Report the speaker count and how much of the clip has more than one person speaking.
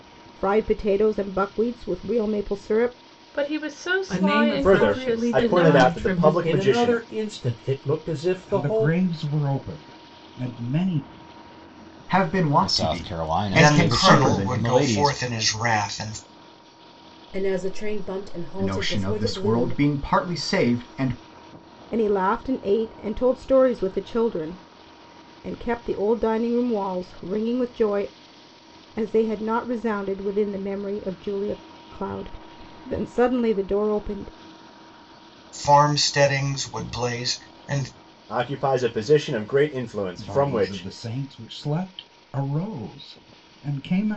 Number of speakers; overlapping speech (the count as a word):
ten, about 18%